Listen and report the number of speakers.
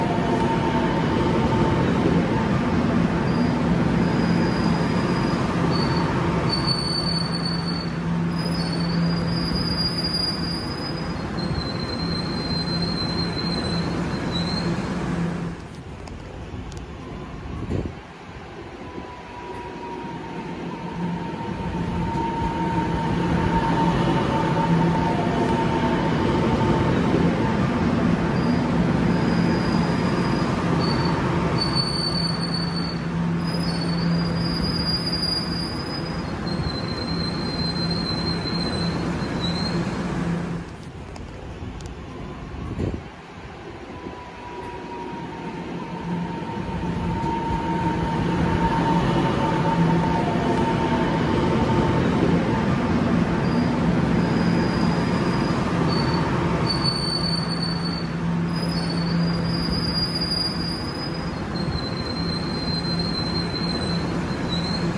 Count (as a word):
zero